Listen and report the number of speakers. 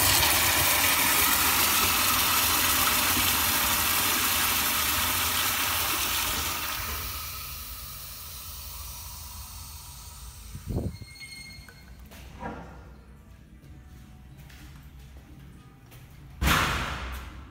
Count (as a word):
zero